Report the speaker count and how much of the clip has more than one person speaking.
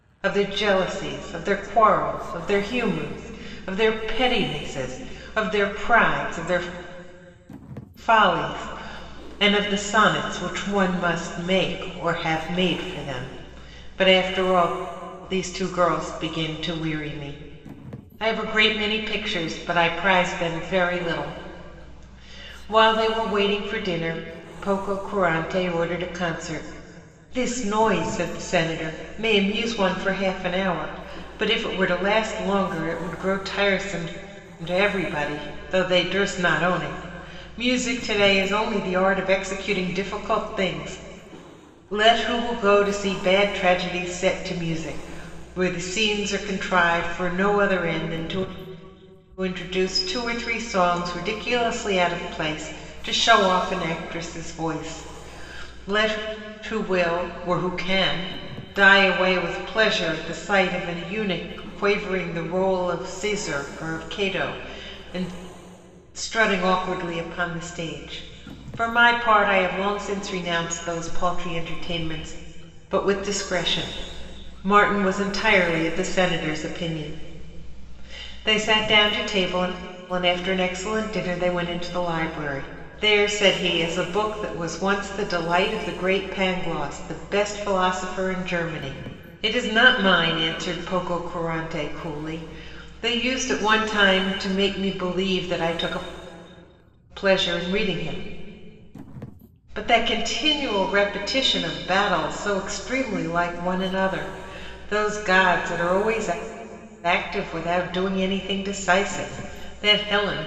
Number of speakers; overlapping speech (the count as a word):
one, no overlap